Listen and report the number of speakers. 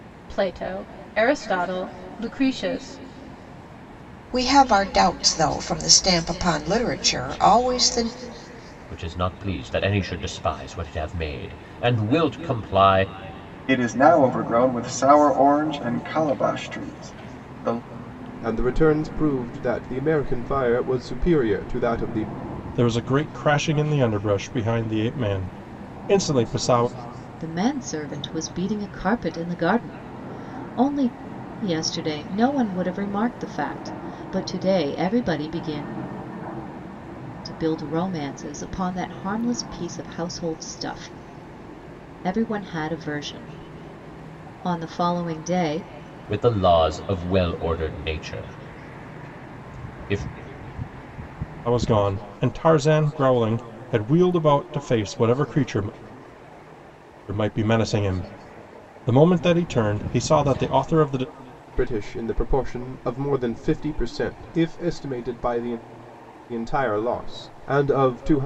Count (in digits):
7